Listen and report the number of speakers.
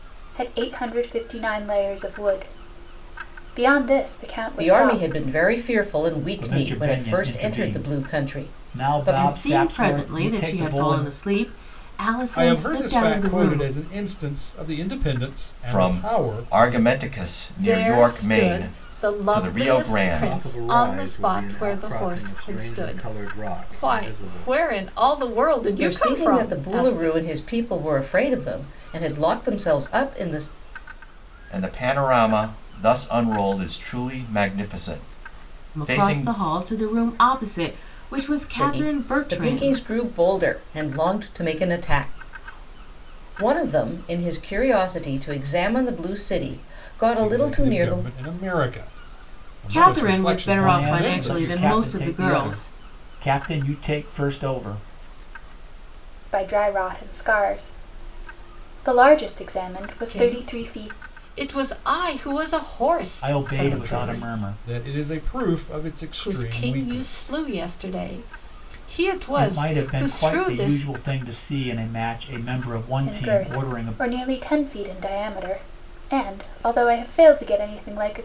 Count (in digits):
8